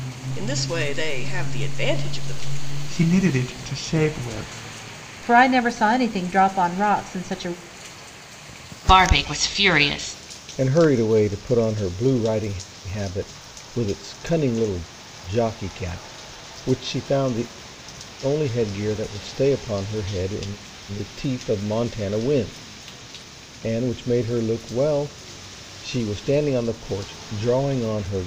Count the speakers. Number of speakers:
five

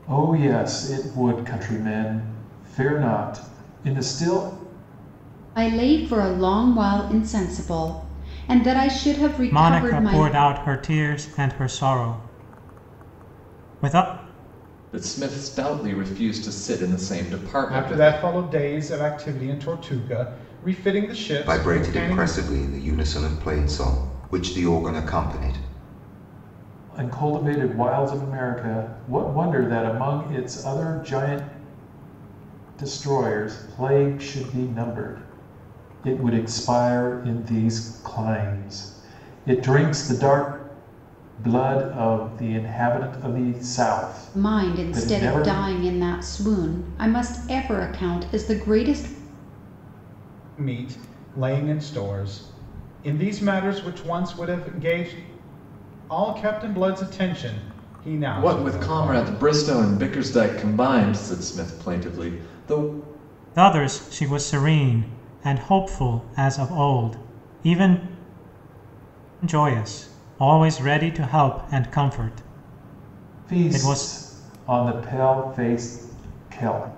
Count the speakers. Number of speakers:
six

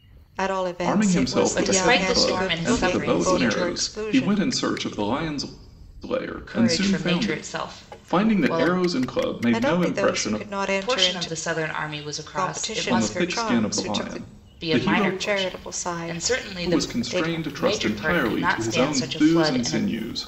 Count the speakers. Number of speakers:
three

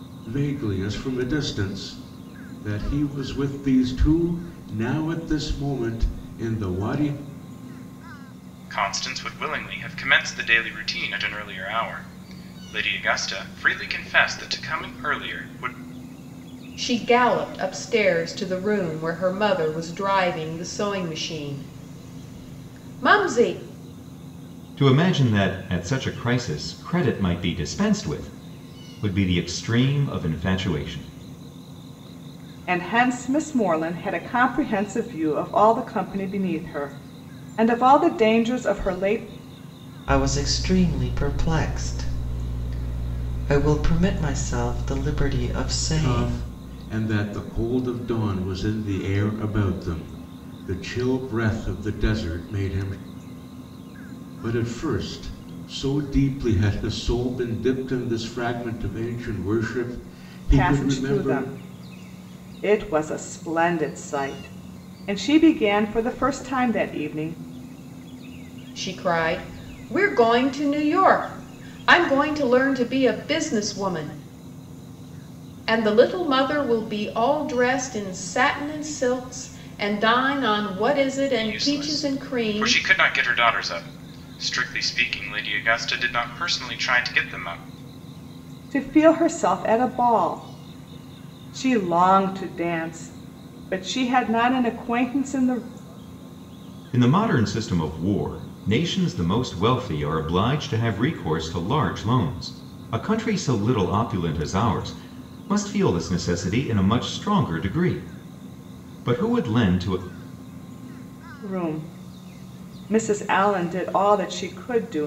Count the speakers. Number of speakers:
six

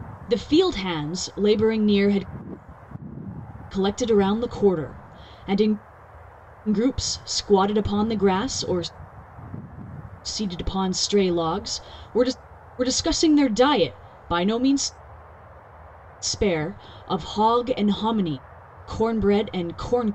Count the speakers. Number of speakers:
one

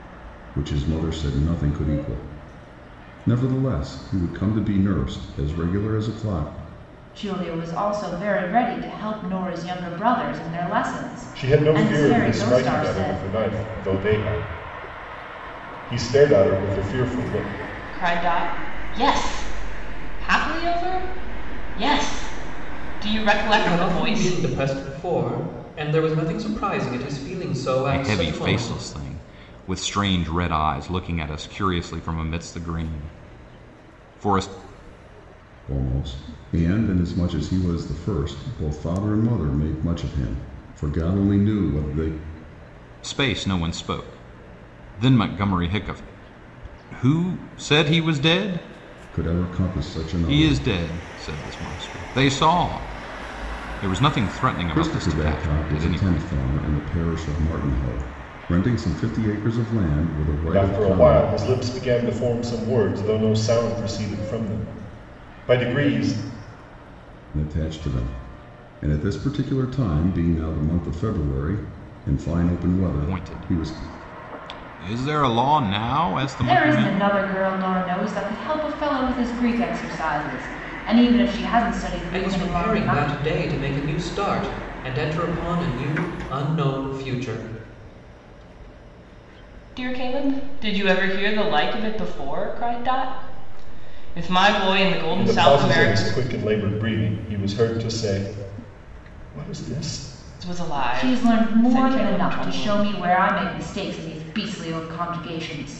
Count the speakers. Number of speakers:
six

